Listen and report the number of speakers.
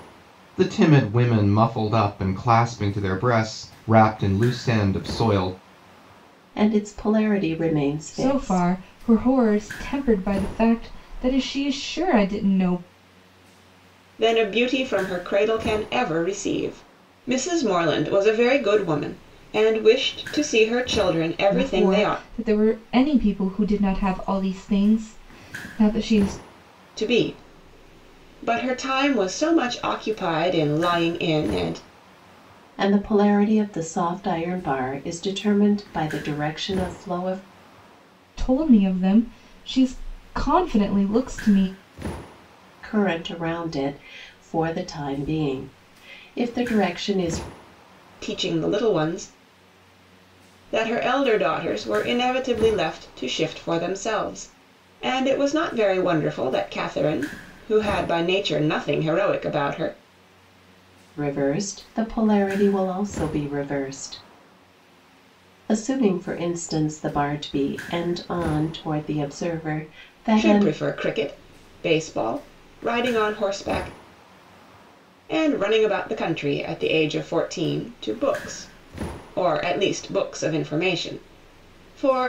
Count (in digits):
4